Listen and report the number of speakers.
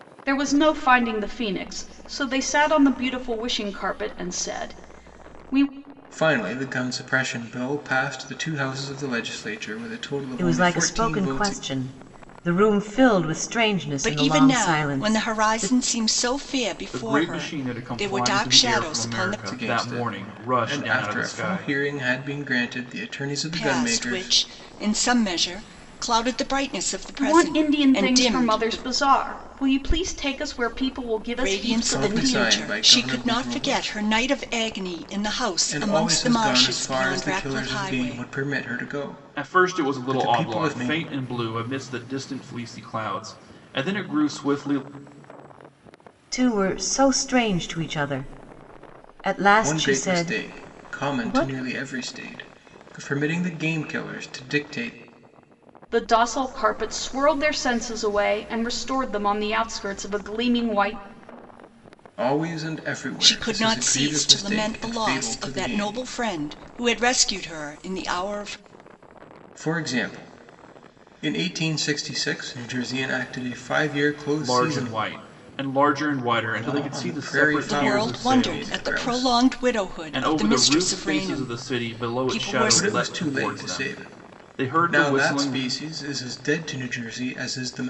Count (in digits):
5